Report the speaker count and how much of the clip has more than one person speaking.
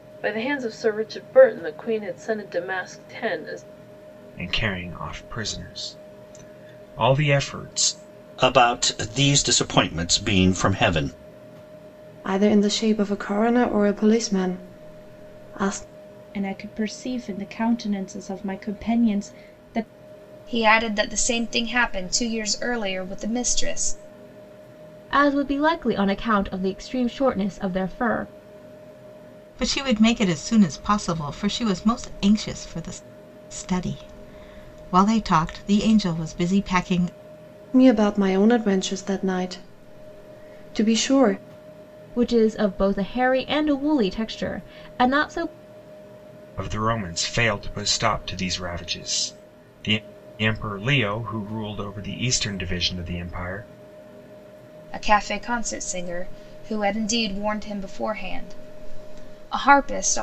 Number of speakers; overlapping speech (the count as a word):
eight, no overlap